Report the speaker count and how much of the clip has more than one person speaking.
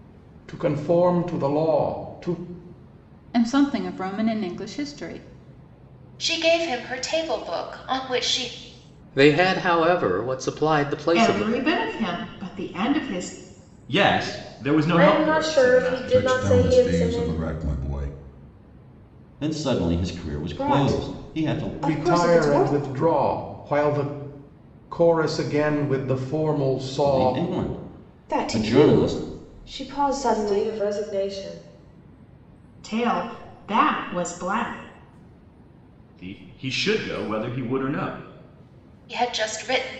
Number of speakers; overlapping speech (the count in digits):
10, about 17%